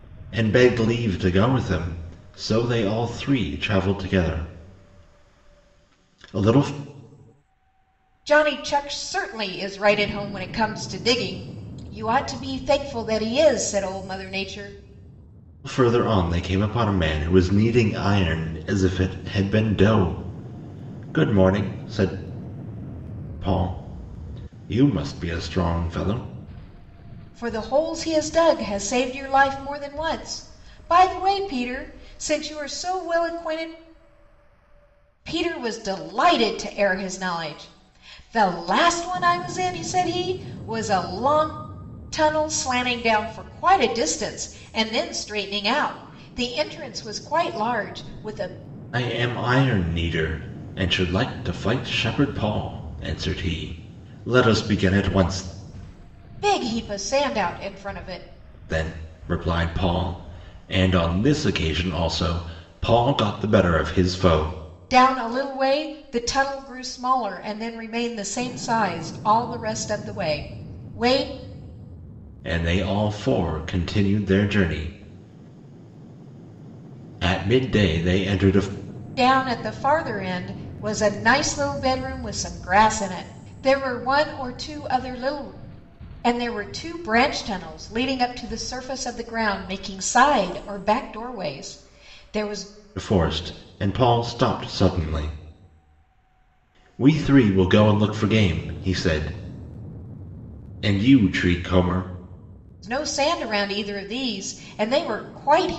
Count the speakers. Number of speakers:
2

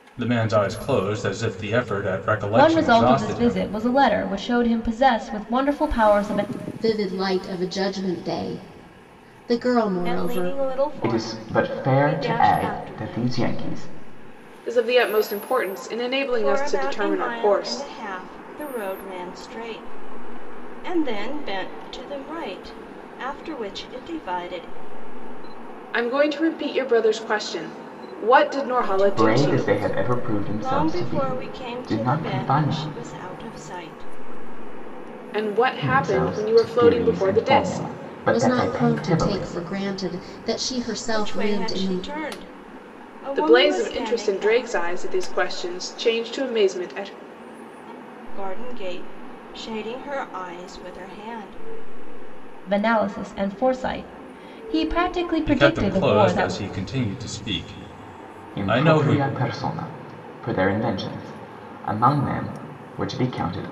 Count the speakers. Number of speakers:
6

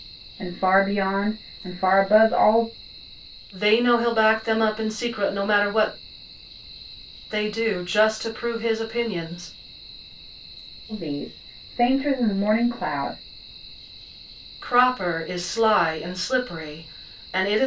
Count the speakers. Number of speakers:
2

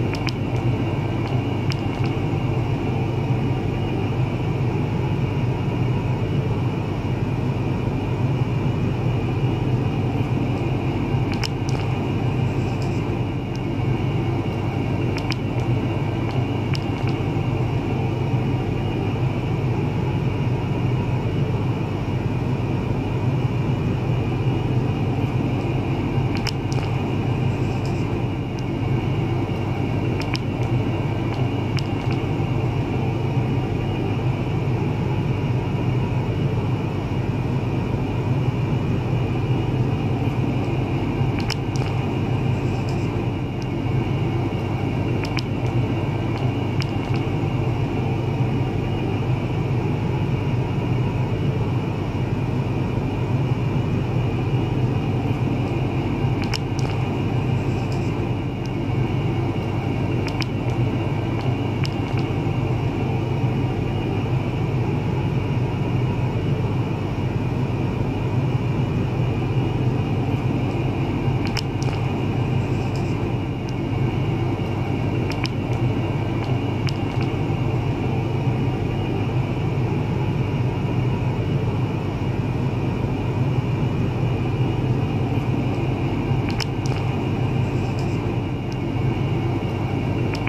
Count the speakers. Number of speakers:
0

